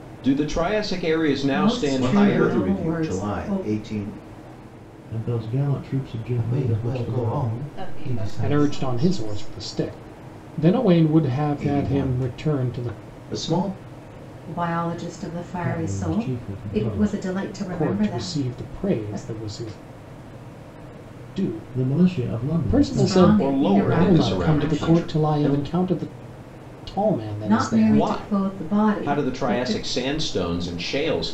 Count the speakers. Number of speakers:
7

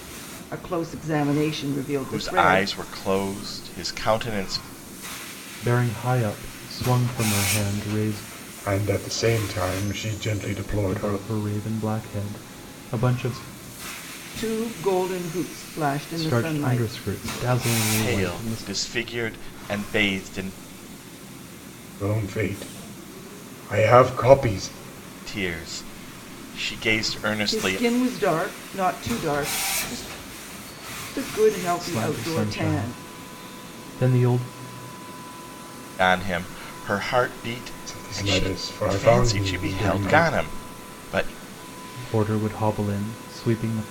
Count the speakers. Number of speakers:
4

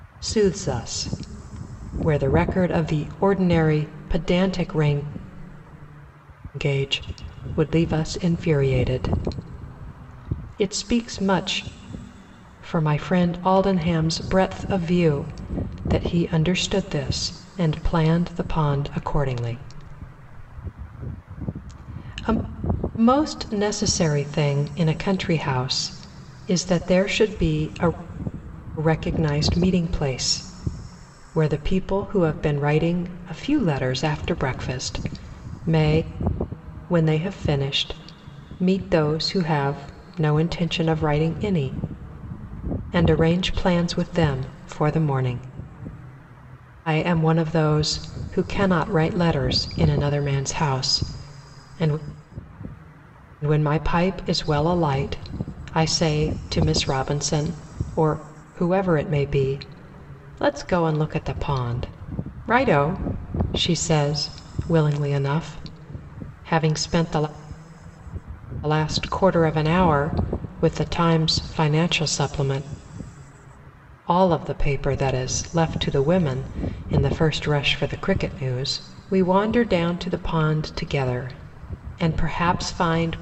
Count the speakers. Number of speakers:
1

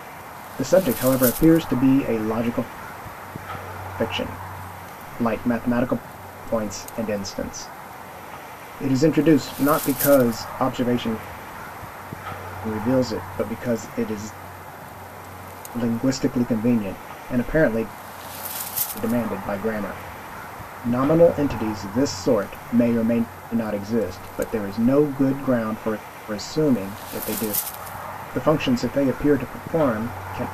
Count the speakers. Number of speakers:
1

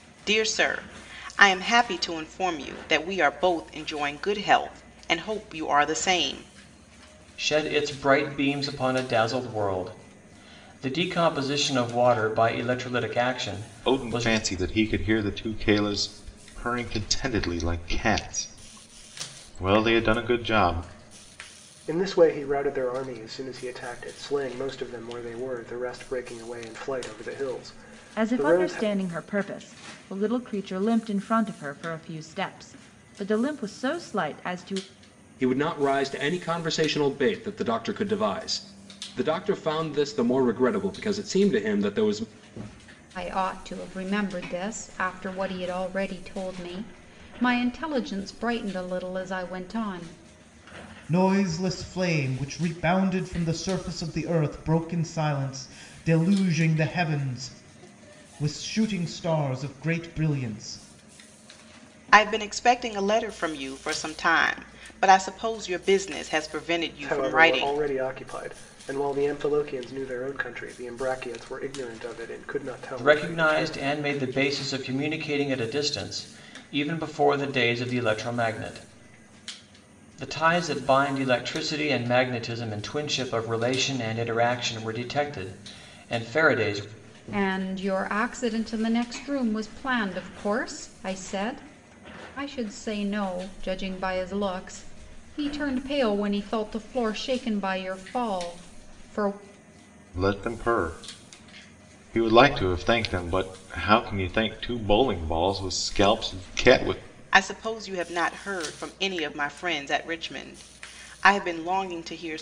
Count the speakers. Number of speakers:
8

